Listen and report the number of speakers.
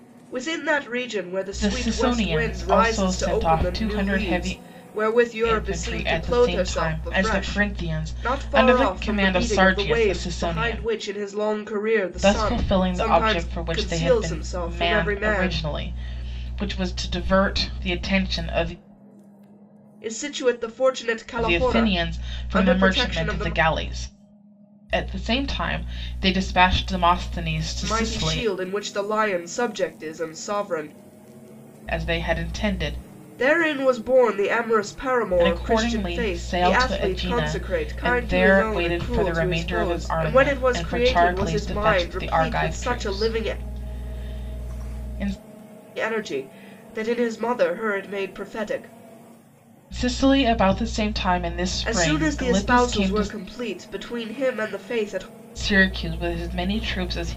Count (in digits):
2